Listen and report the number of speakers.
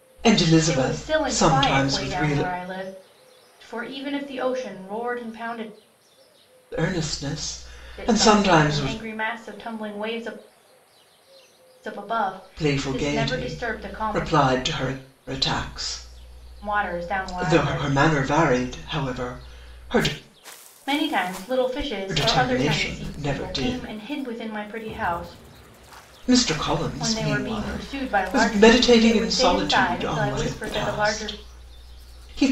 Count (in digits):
2